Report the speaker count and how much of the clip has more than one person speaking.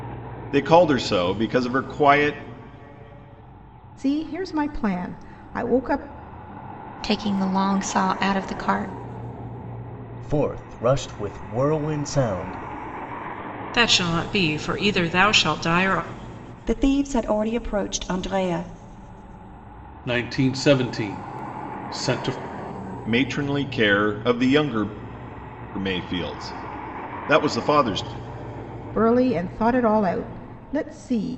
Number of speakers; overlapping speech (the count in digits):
7, no overlap